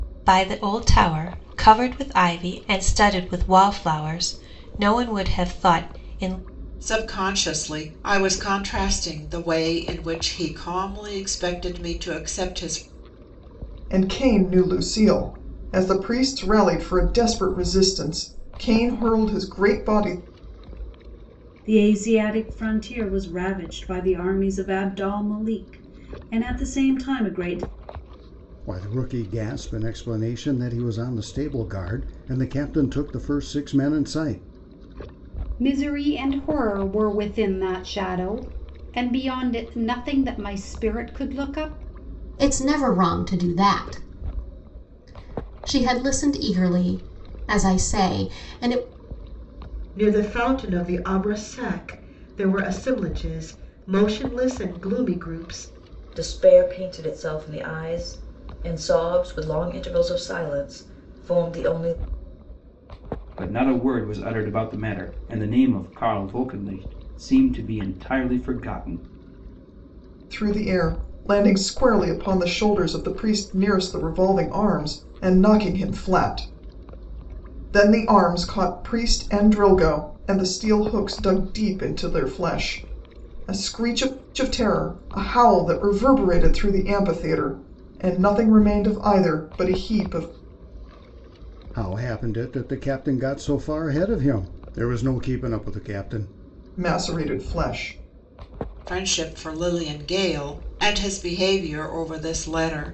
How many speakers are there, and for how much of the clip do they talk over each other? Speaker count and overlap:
10, no overlap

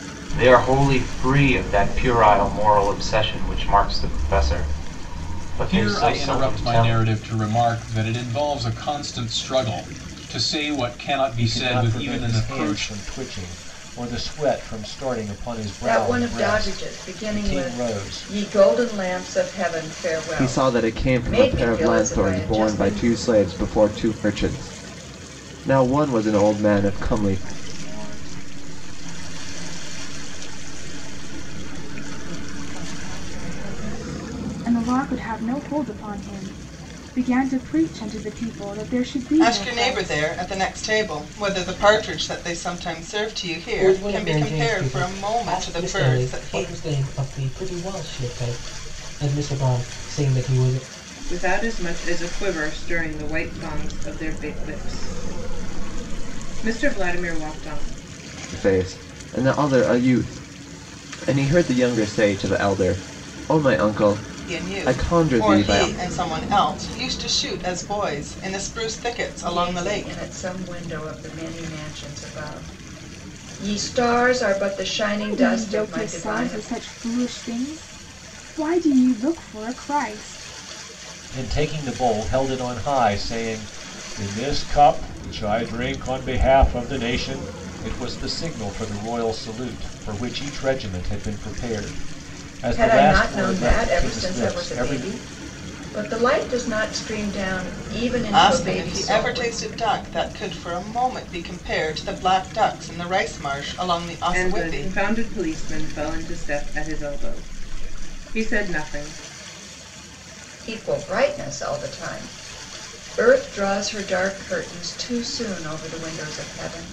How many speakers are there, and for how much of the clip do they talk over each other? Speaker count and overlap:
10, about 18%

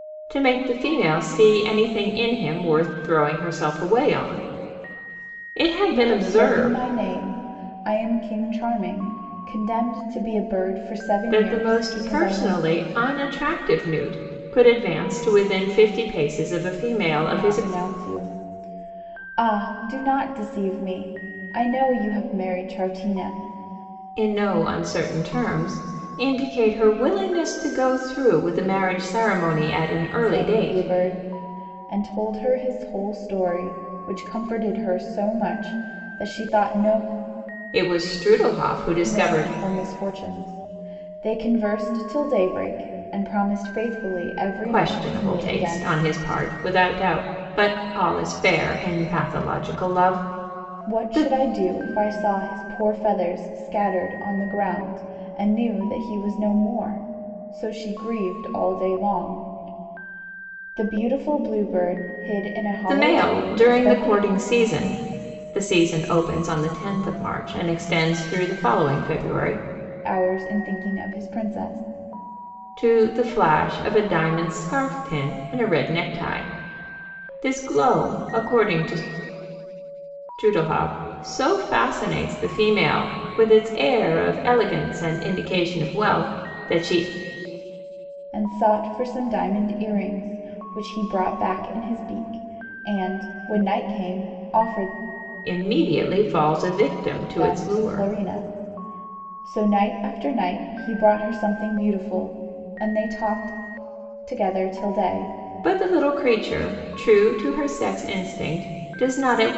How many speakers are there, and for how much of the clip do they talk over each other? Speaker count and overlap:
2, about 7%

